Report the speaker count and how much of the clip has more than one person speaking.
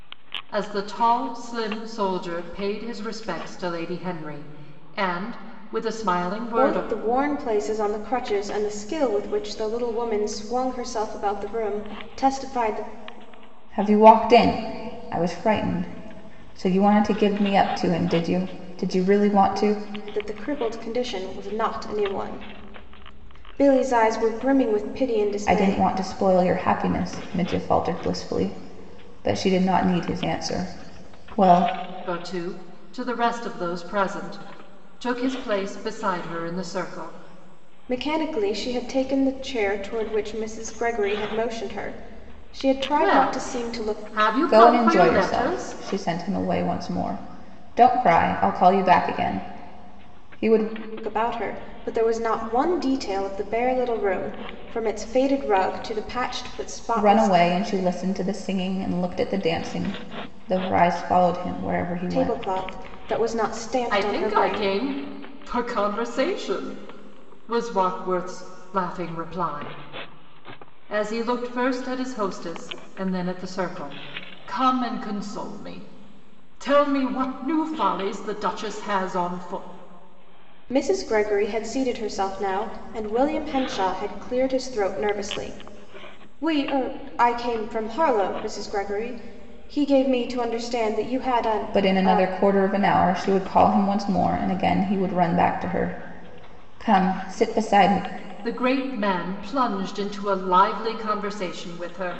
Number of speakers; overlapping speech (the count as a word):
three, about 5%